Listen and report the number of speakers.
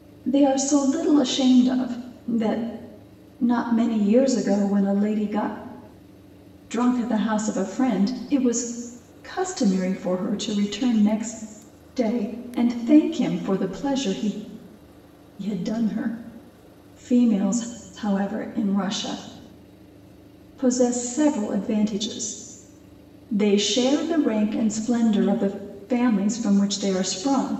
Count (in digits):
1